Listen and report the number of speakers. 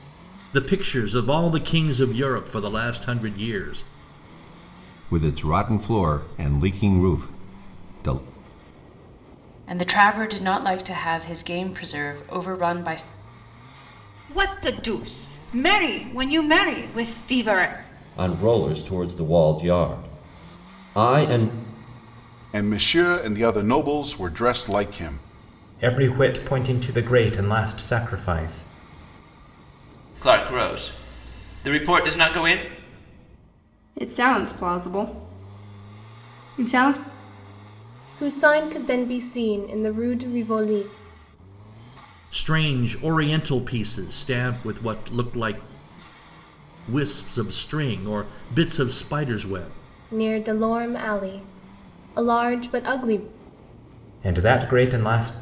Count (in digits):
10